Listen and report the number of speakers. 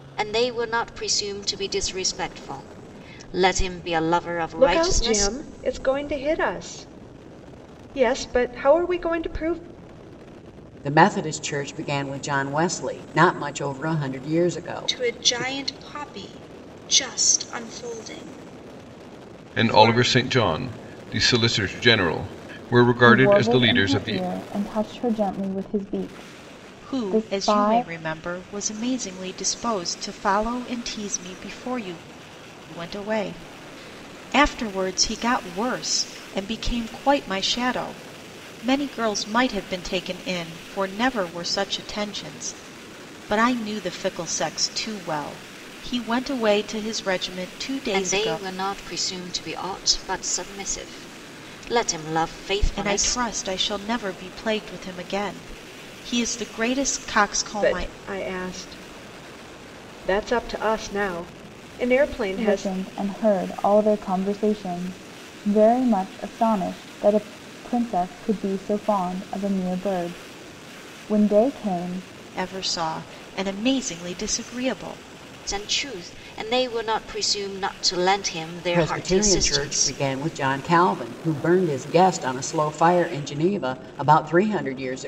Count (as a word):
seven